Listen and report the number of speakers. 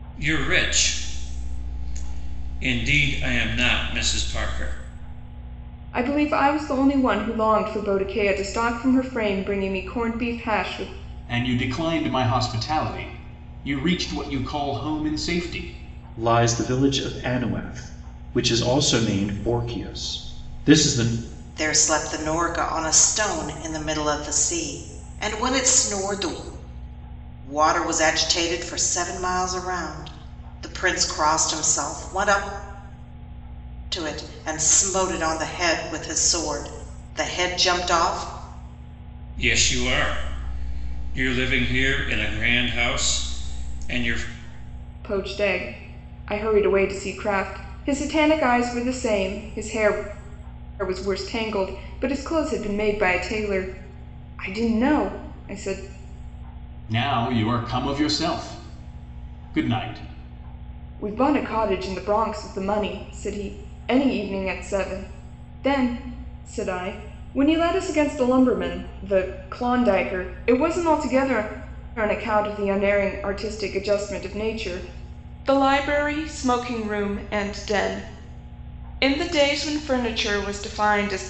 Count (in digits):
5